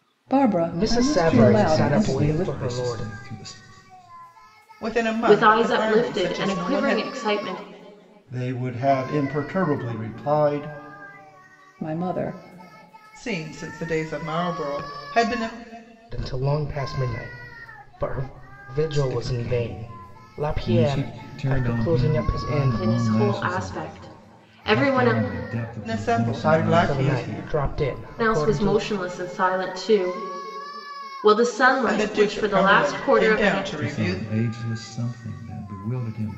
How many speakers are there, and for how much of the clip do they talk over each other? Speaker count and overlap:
6, about 38%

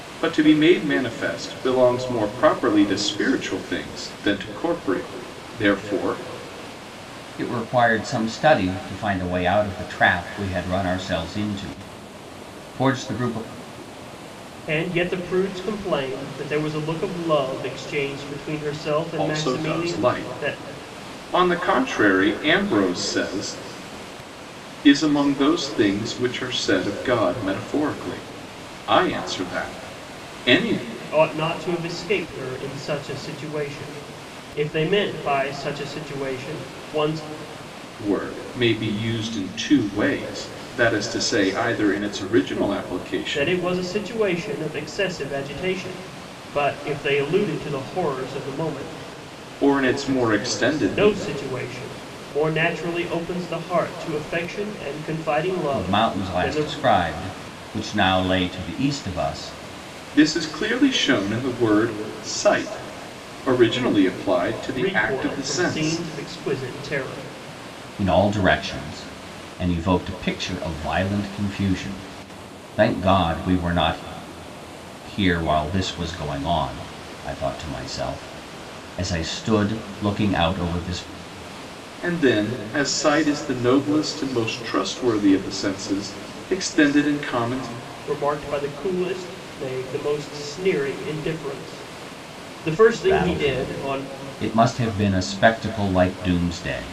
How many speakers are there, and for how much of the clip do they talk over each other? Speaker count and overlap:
3, about 6%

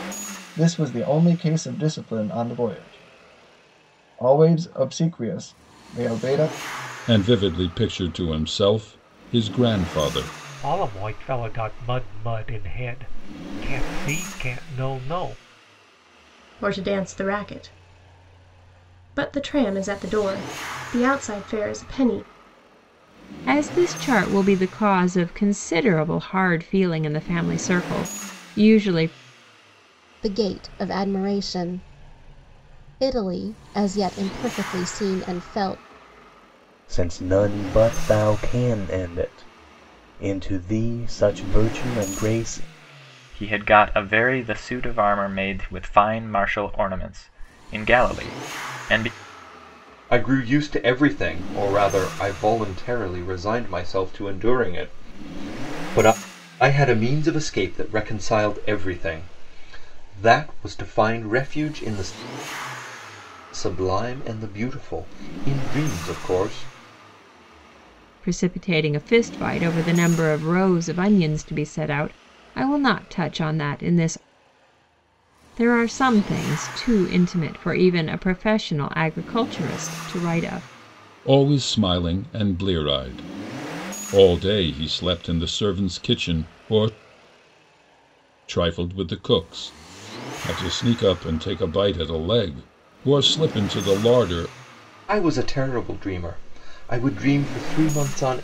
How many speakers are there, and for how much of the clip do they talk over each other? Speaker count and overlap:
9, no overlap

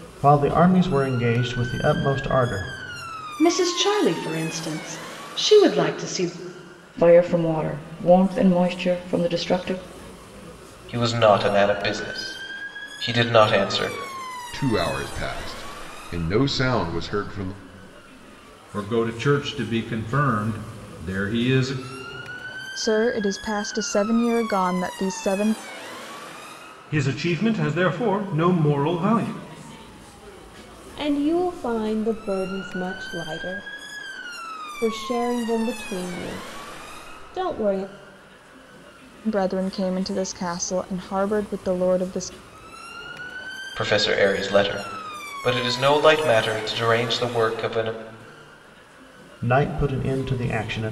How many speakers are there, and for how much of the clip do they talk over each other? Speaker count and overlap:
9, no overlap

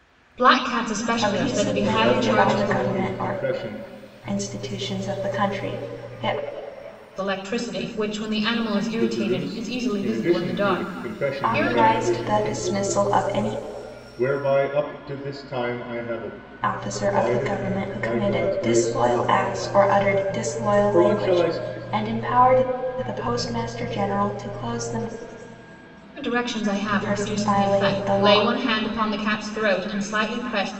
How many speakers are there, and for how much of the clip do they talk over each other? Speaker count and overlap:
3, about 41%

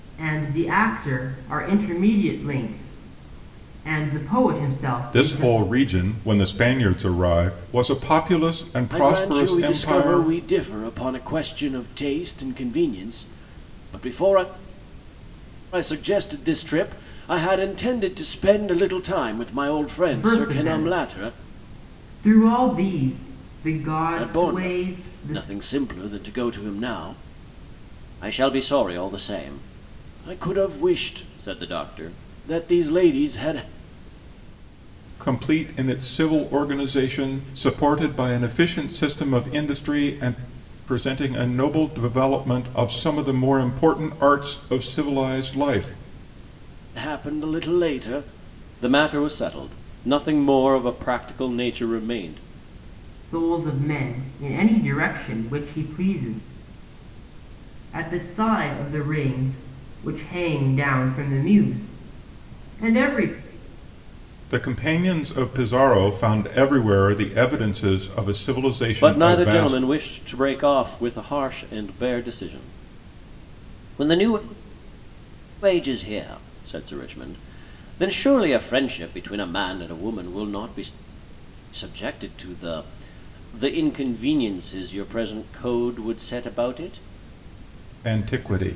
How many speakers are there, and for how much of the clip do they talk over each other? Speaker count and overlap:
3, about 6%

